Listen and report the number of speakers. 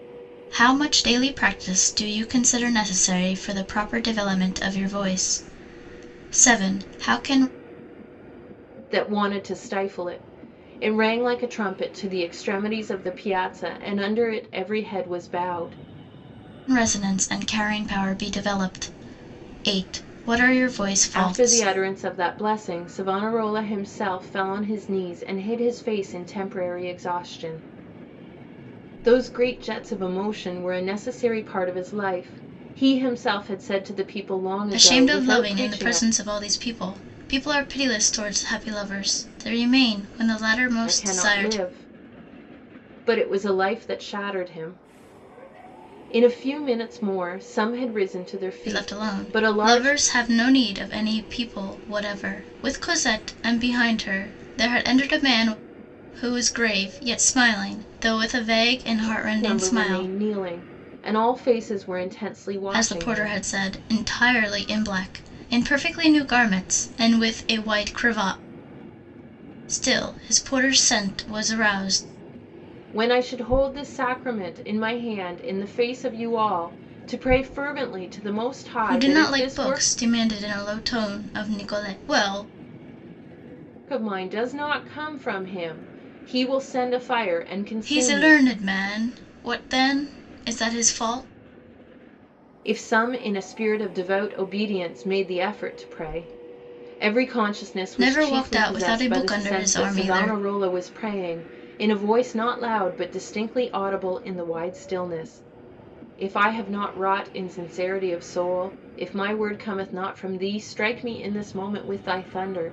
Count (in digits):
2